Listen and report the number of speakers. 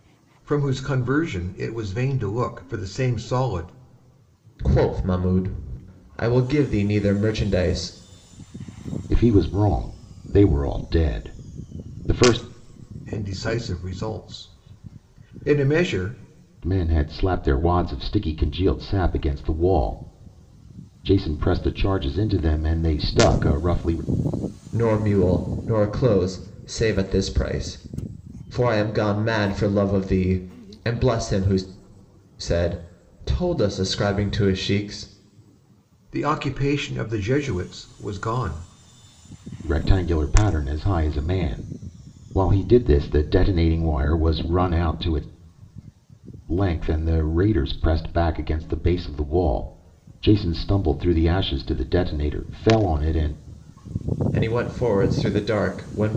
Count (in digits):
3